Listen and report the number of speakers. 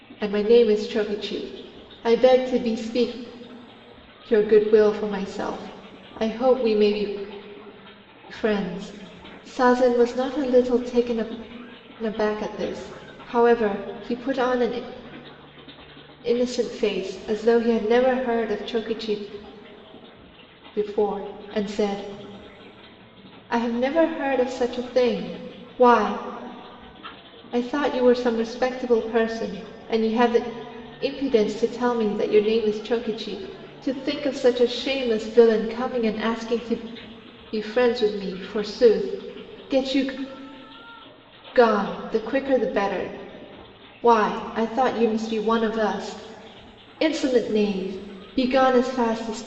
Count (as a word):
one